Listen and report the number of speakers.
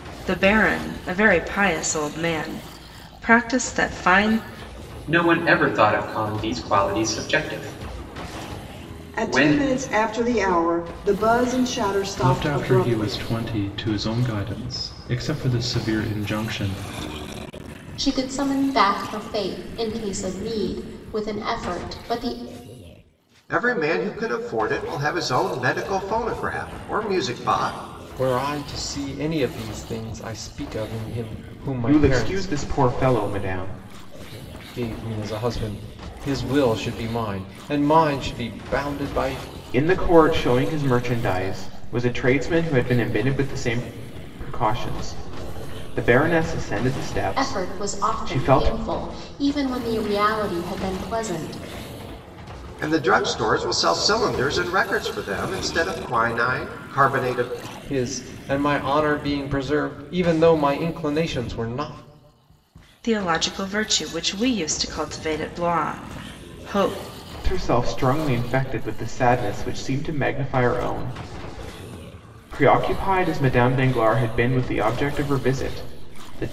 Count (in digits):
8